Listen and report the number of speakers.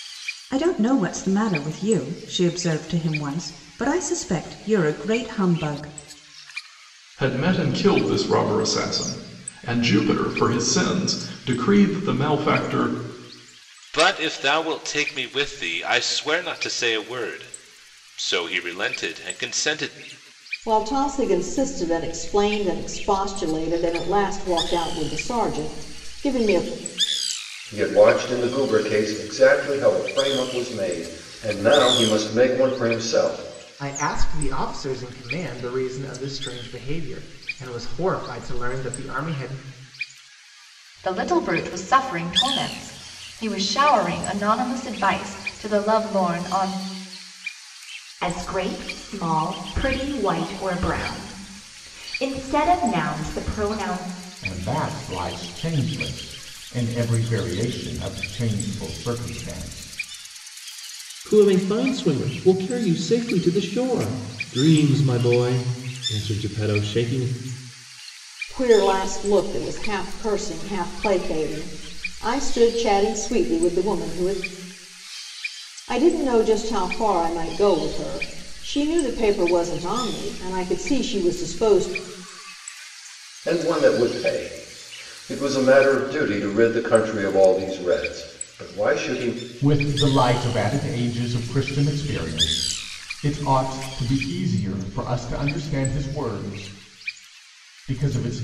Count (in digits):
10